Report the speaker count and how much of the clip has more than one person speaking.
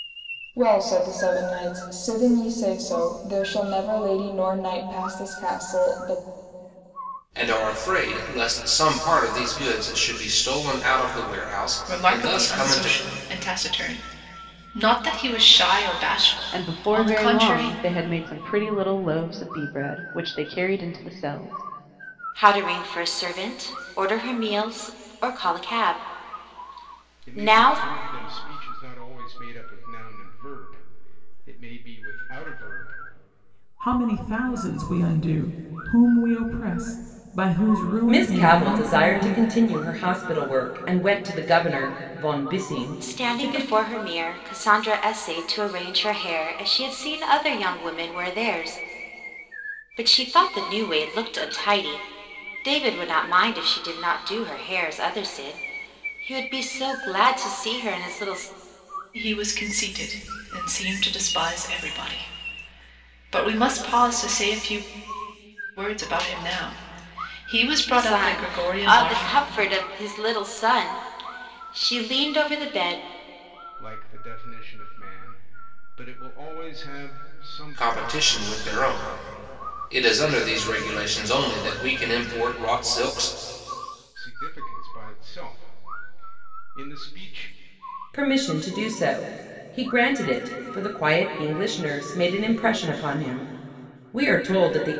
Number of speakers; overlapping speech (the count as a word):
eight, about 8%